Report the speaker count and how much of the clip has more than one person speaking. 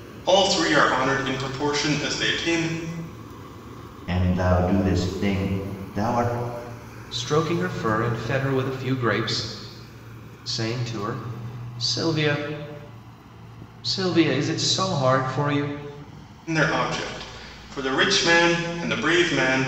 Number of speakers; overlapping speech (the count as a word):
three, no overlap